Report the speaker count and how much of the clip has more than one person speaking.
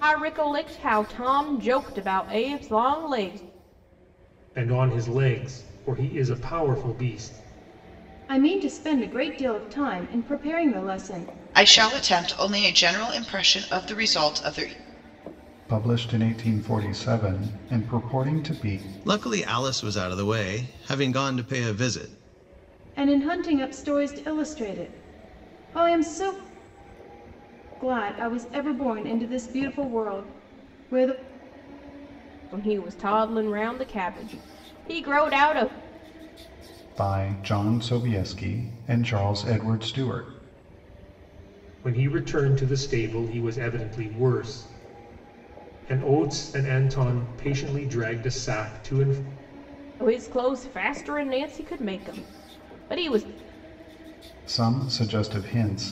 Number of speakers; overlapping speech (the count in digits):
6, no overlap